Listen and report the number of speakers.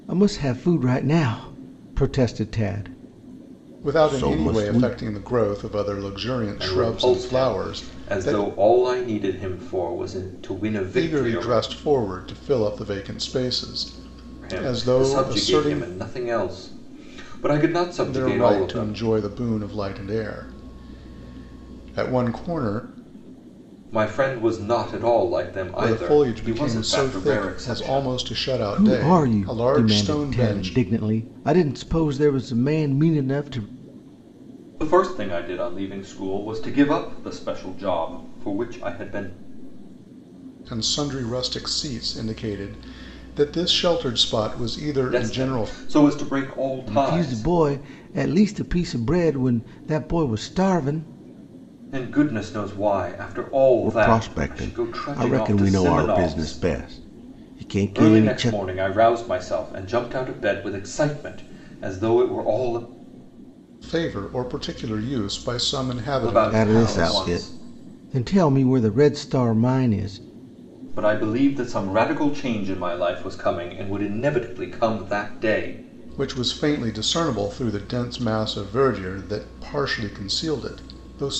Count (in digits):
3